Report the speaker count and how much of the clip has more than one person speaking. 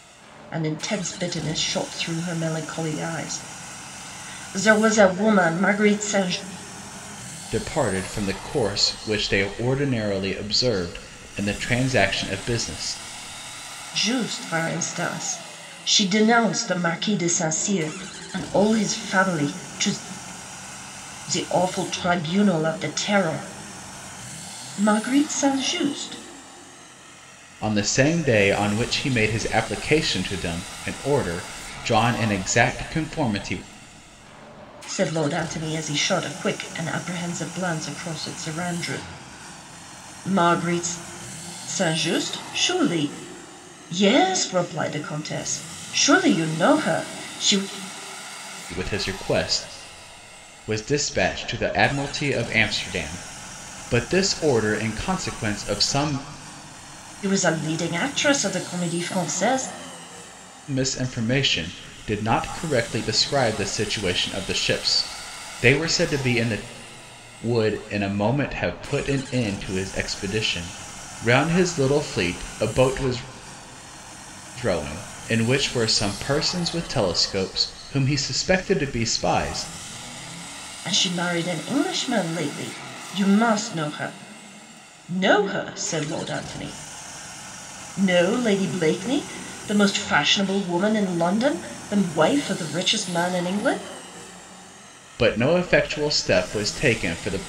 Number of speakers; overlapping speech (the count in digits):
2, no overlap